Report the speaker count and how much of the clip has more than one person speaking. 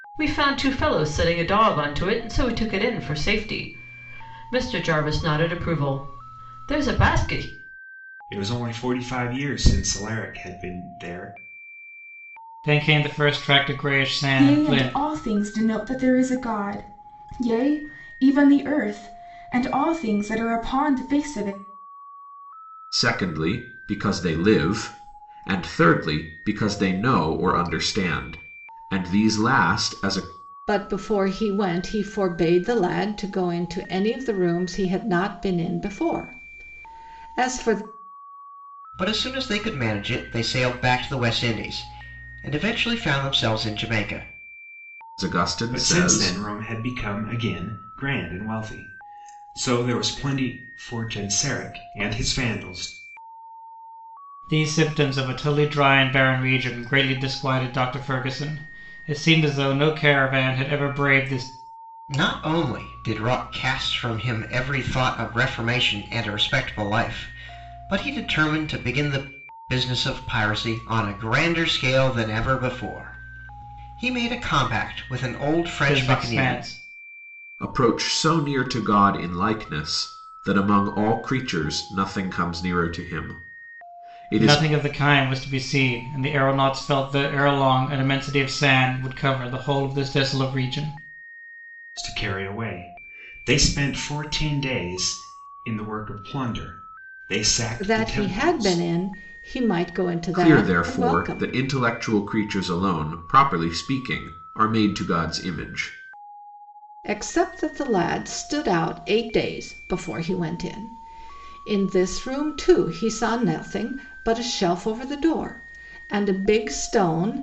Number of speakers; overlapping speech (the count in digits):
7, about 4%